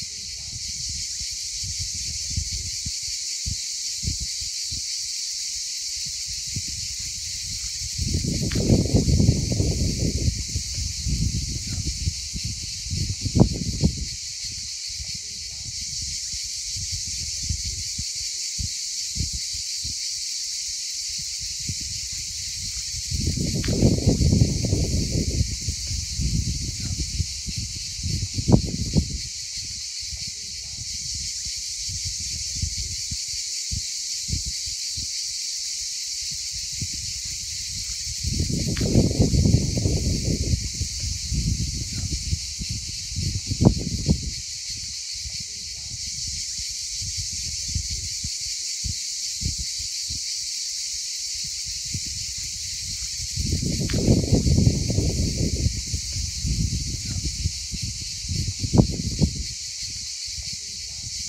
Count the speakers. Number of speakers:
zero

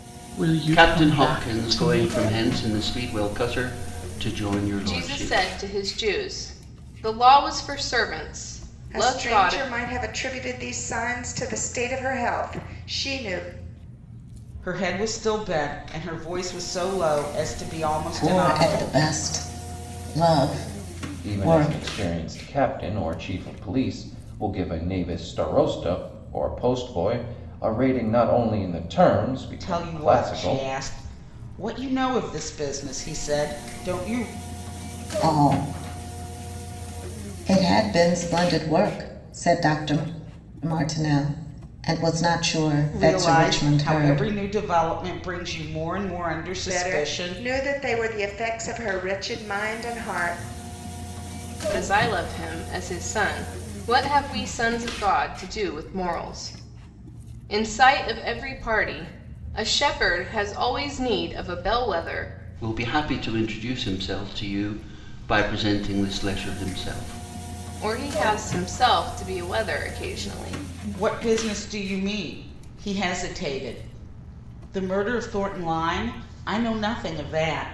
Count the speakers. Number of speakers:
seven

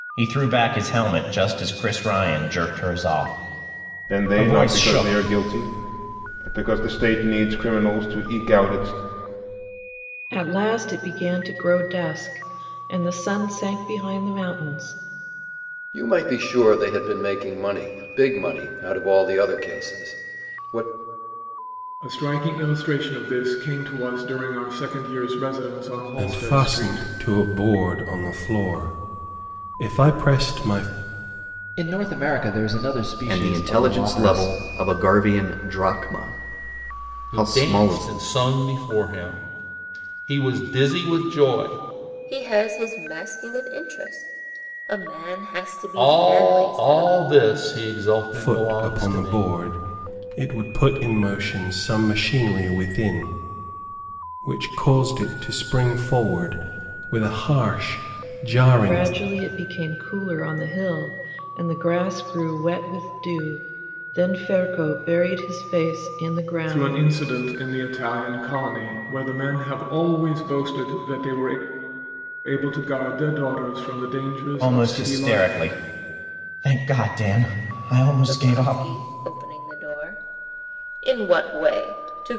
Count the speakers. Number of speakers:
ten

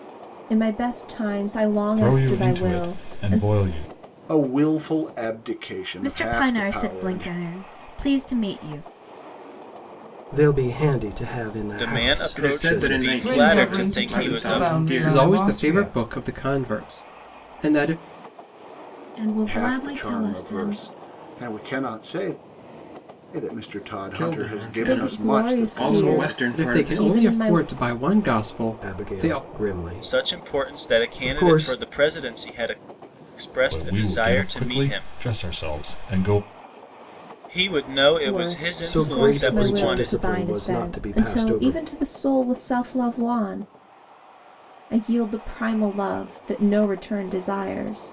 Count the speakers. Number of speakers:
ten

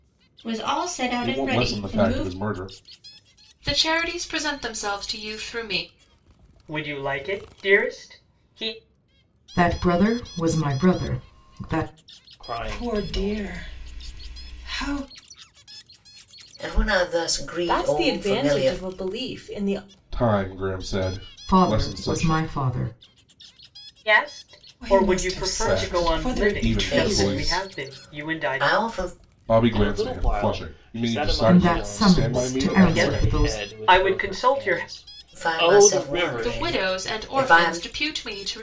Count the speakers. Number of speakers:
nine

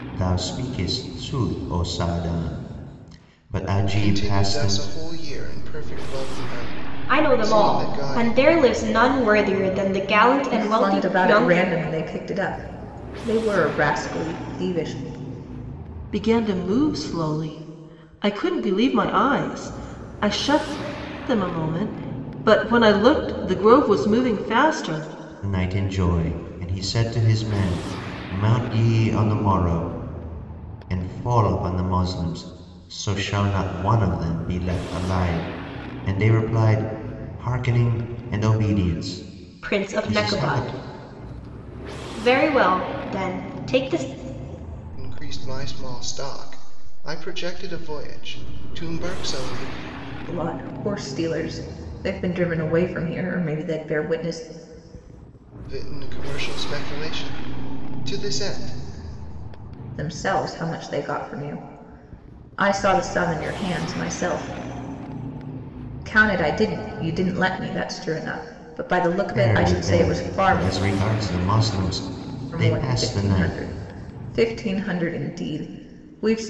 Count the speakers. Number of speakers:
five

